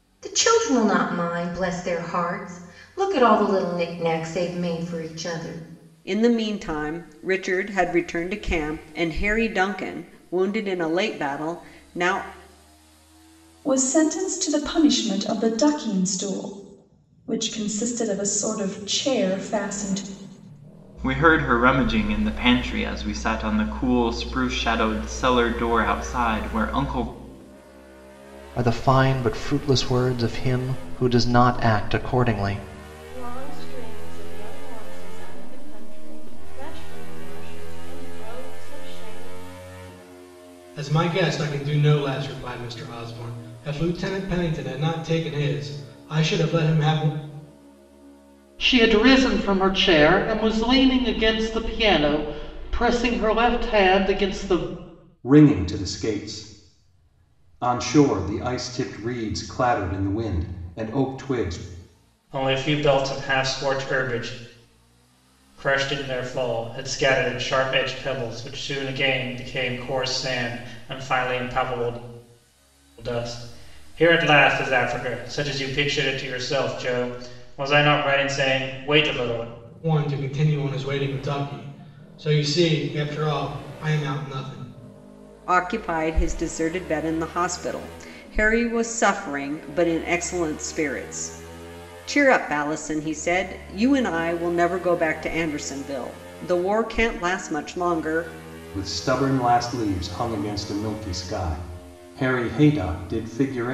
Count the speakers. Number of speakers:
ten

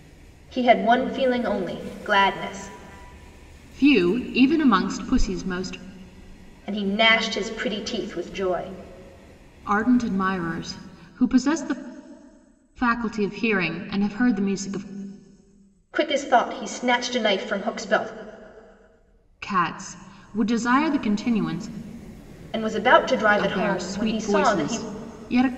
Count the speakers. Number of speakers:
two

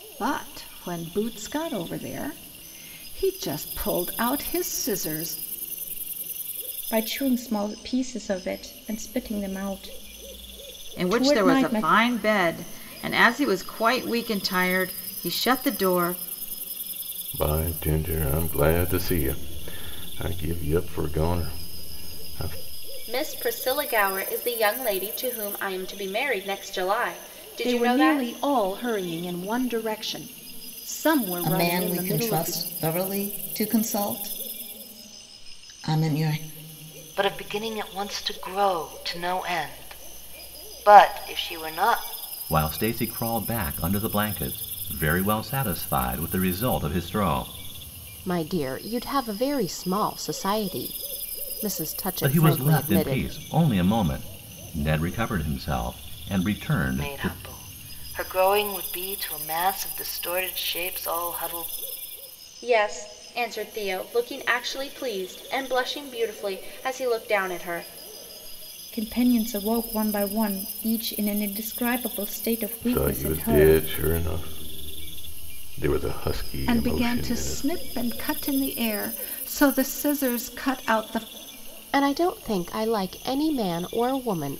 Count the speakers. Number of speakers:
ten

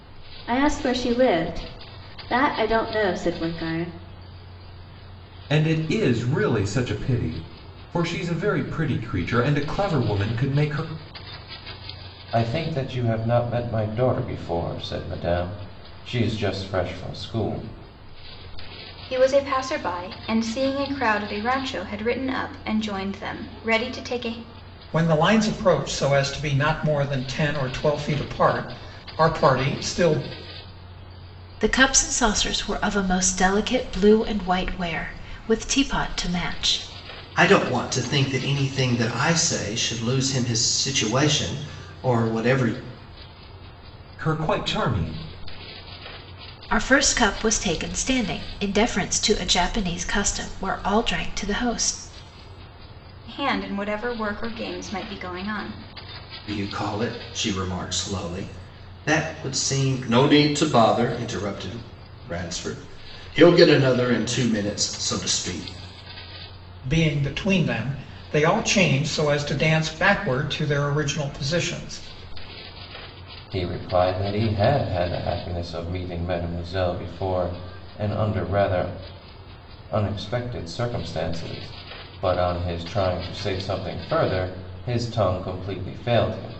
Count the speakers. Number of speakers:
seven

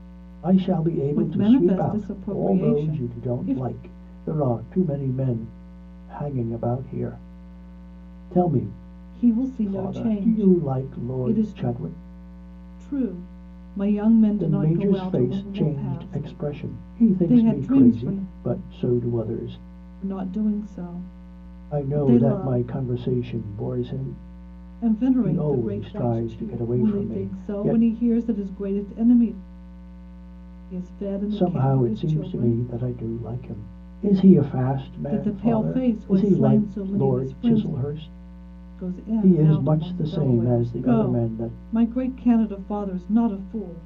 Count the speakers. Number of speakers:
two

